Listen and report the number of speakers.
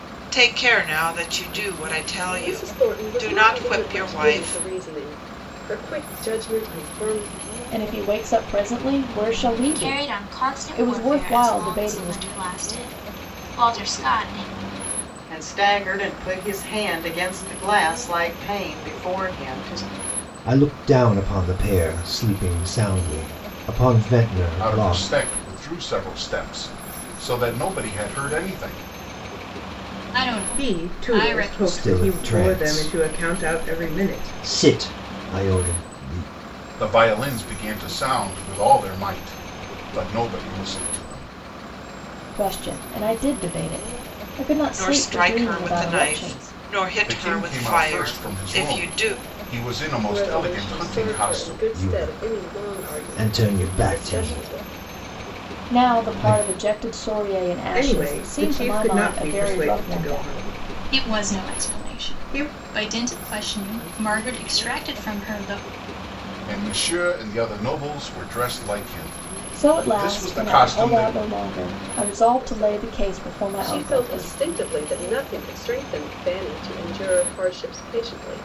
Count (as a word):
nine